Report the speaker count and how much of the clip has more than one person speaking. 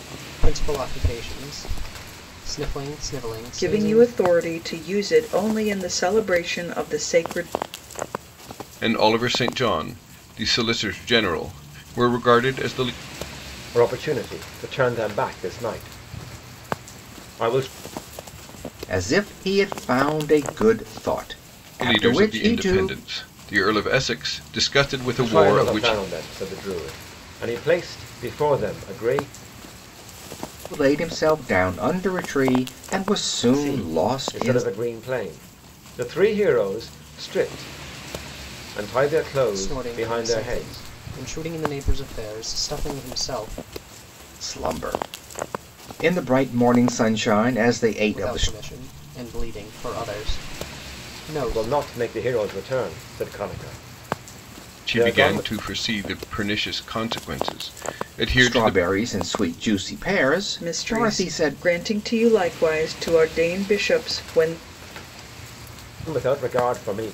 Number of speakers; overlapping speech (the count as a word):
five, about 12%